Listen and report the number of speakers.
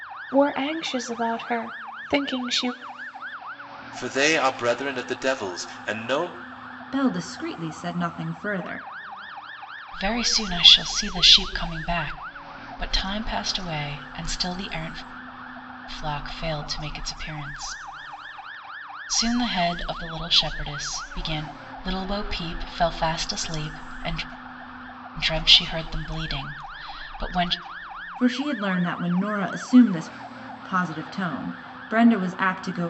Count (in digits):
4